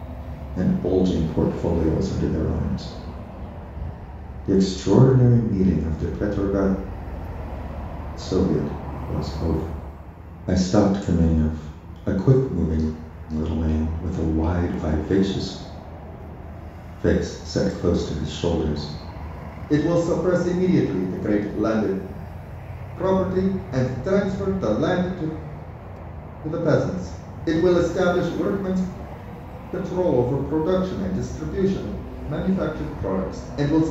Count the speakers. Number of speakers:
1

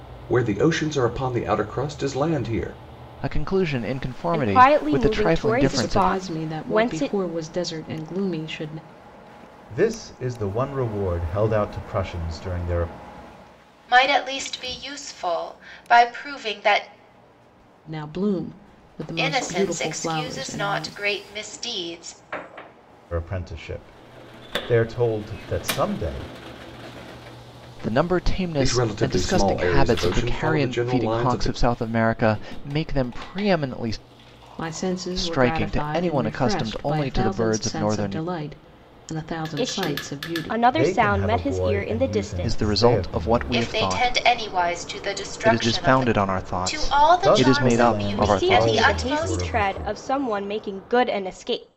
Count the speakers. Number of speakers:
6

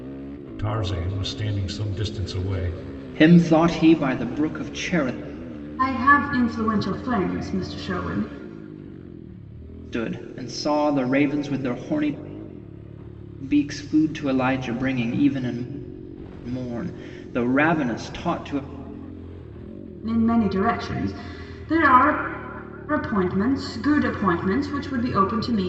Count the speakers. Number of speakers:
3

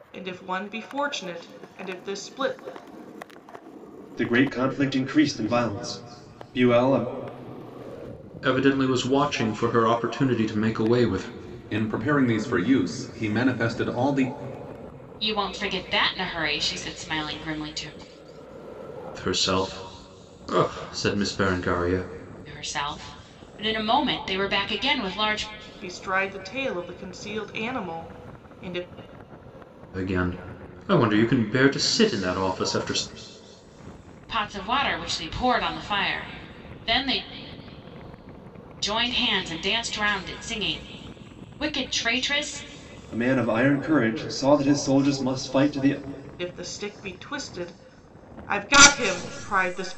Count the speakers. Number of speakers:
5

